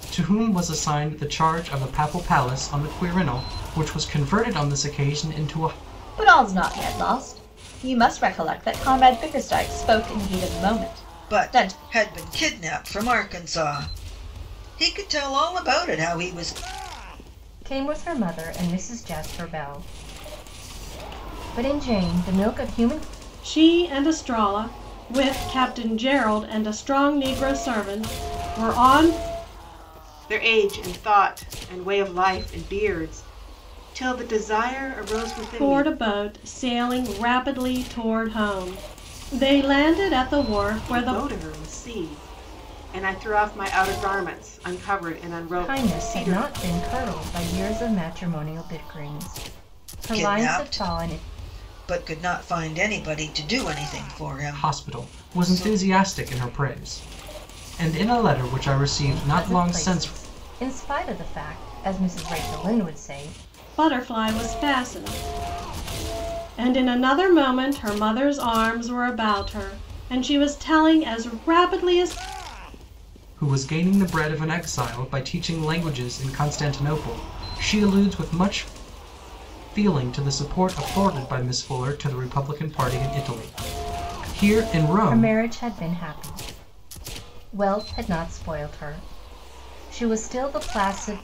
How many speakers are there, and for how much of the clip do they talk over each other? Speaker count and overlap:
6, about 6%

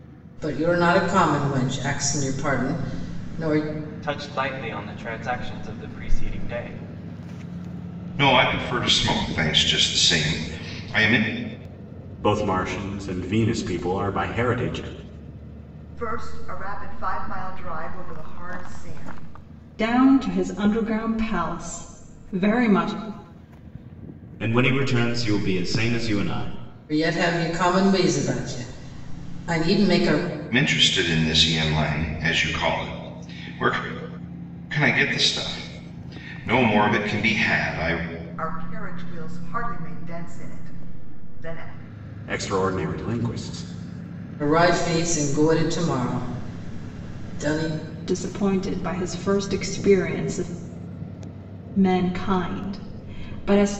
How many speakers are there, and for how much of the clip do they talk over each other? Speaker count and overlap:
7, no overlap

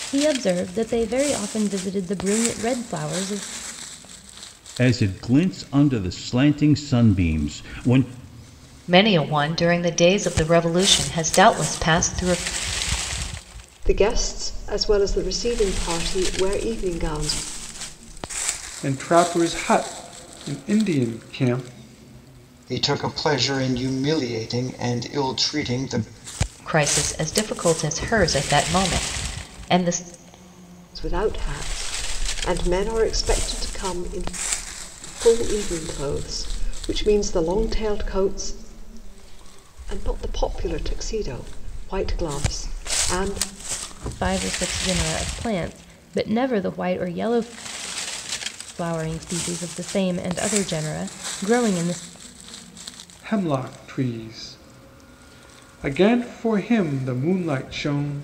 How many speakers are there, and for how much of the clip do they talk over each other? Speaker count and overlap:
6, no overlap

